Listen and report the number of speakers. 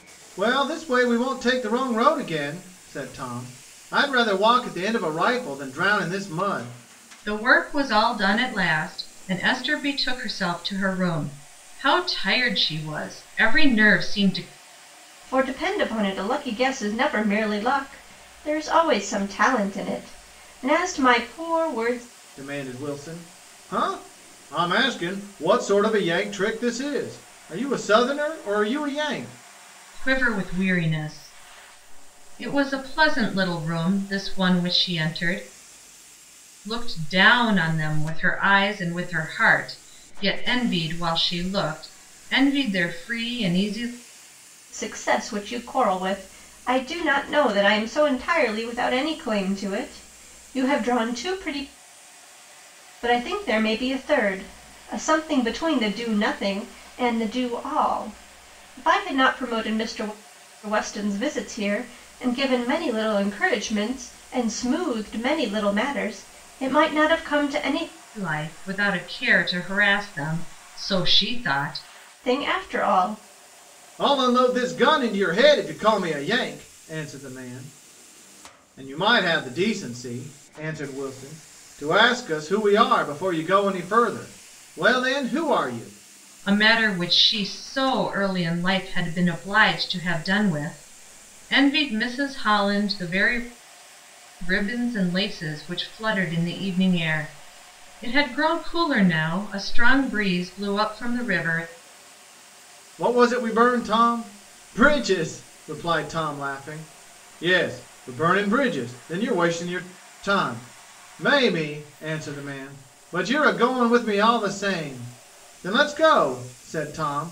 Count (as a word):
three